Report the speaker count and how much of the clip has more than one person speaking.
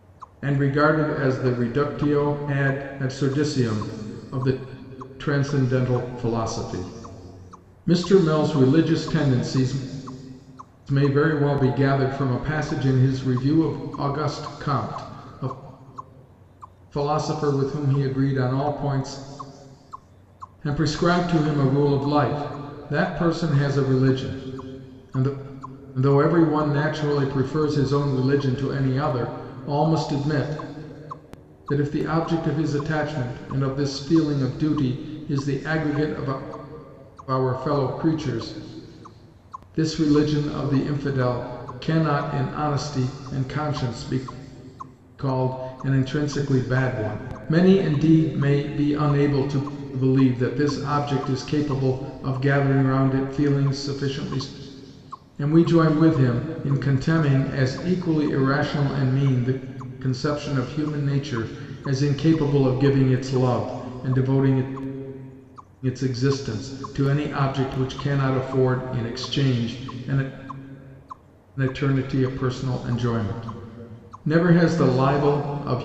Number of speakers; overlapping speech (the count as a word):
one, no overlap